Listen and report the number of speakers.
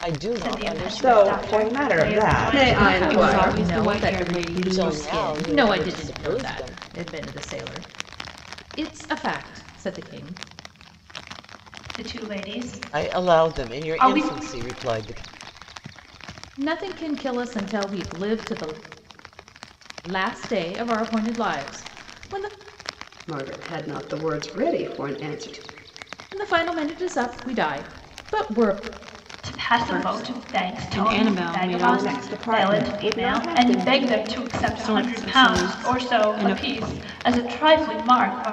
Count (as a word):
six